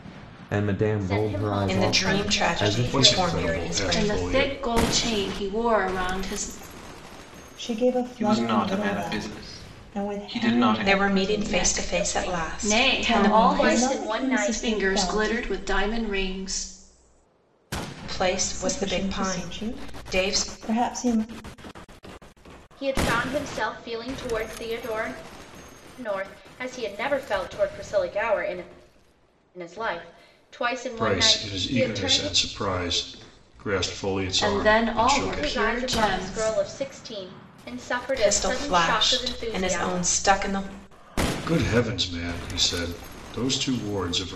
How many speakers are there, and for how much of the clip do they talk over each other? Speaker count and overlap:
seven, about 42%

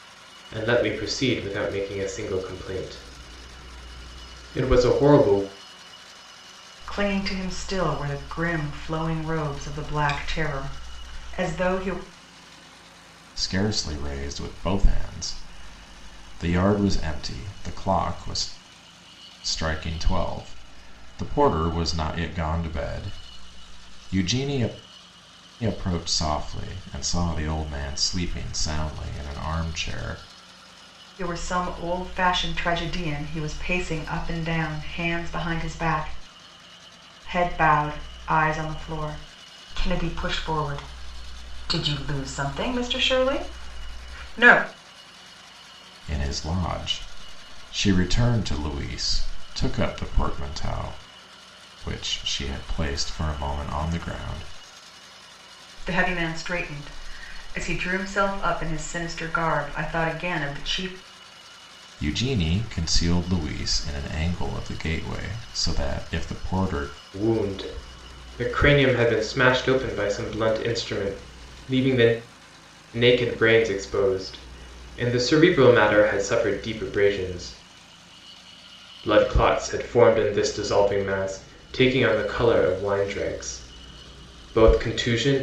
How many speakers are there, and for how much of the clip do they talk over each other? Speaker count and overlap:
three, no overlap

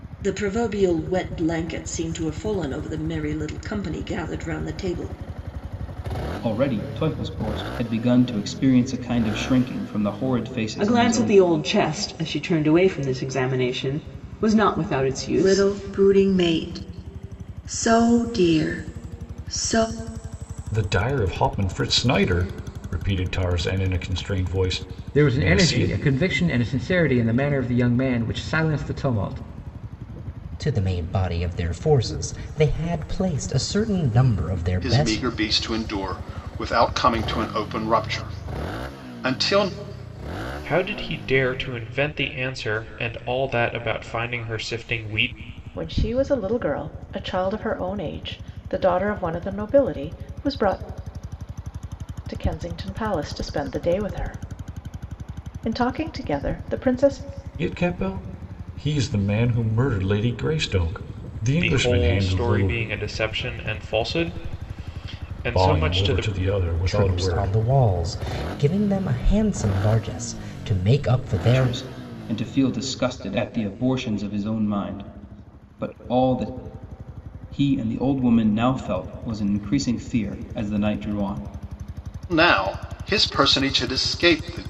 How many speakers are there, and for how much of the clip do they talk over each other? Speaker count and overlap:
ten, about 7%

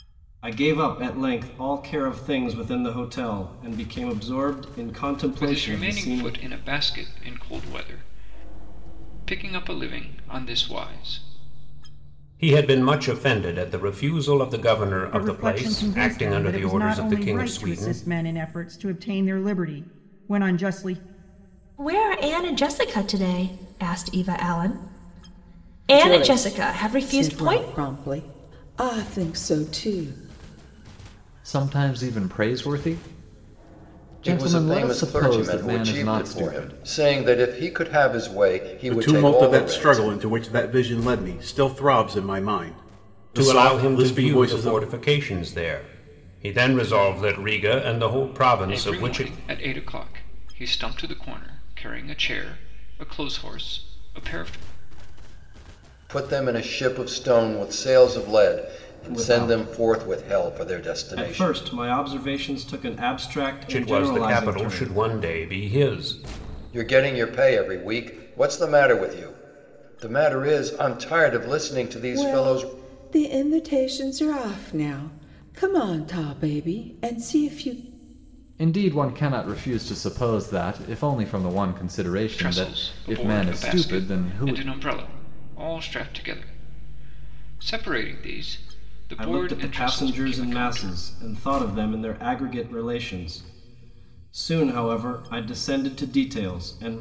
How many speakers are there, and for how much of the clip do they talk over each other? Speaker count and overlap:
nine, about 21%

